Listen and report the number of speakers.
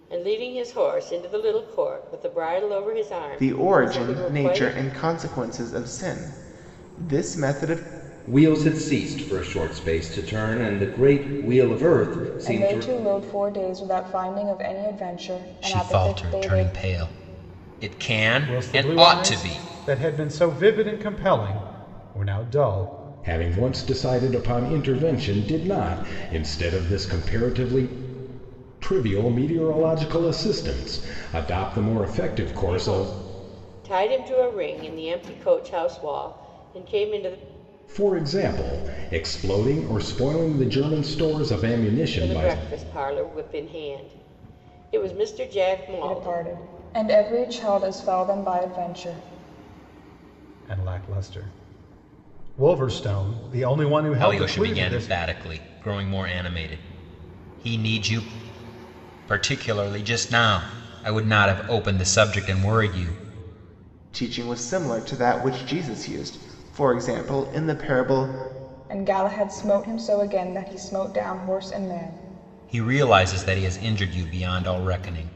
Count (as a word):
seven